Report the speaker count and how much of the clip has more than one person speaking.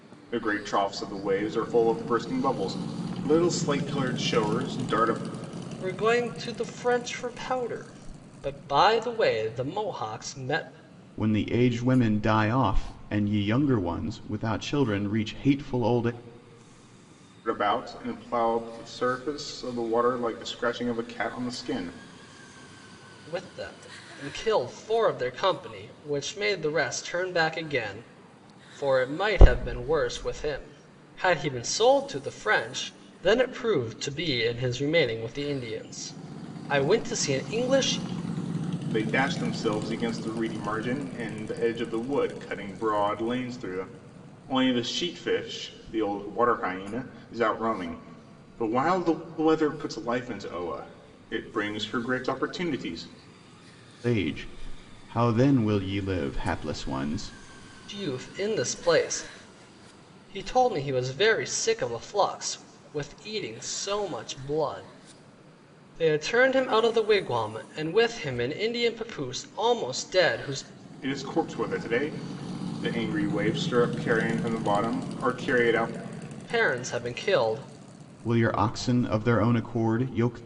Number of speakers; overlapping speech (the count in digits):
3, no overlap